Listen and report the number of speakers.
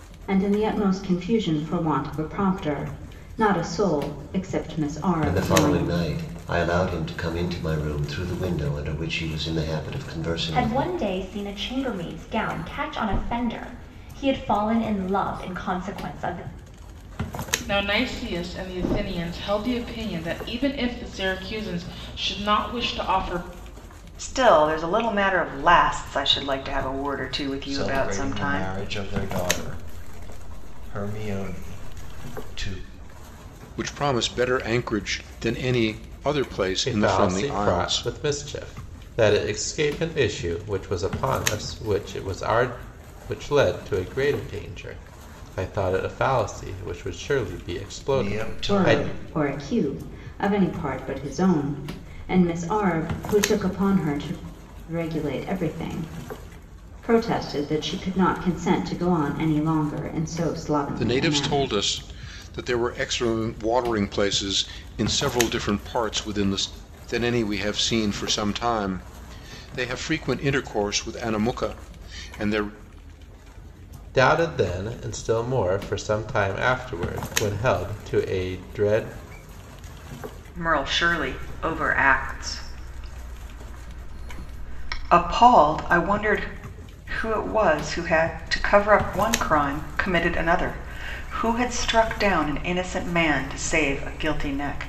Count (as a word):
eight